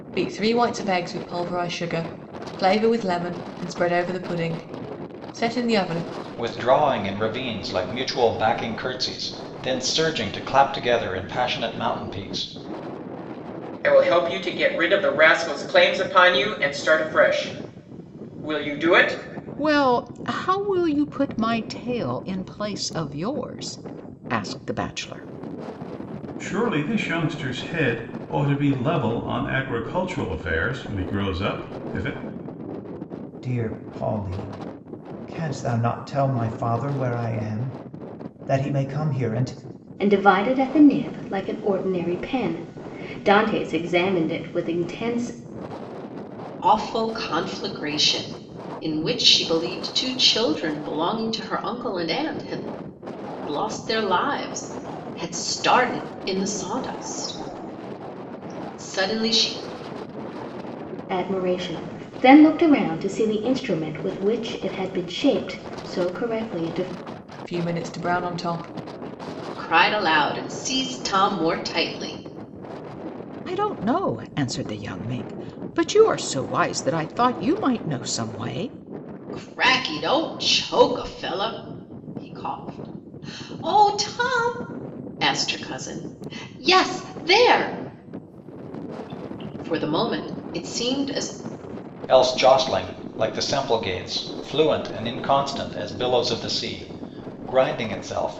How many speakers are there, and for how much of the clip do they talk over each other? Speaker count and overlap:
eight, no overlap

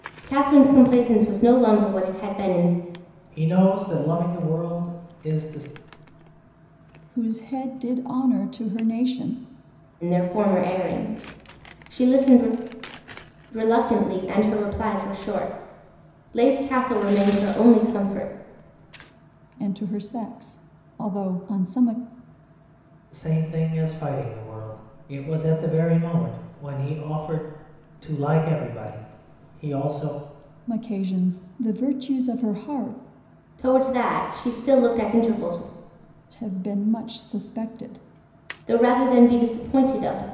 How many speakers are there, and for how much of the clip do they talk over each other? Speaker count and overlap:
three, no overlap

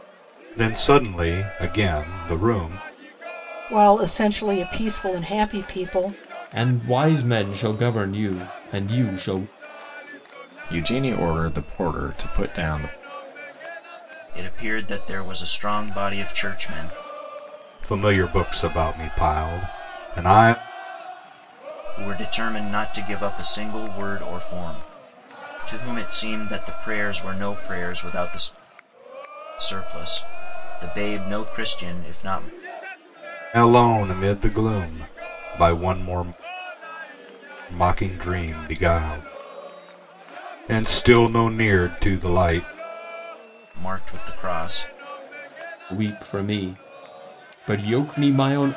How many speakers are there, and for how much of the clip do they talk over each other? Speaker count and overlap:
five, no overlap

